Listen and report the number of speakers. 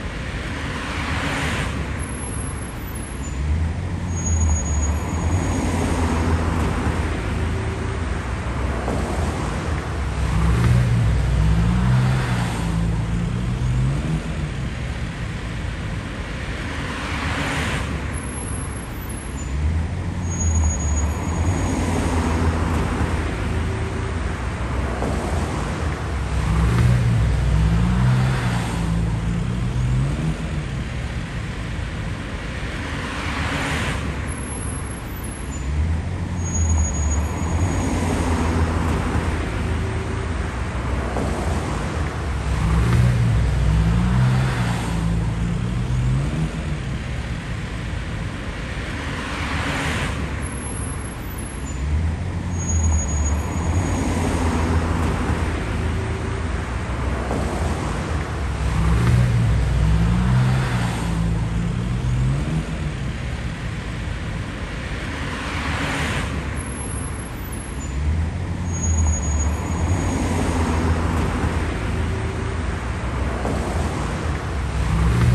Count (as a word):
zero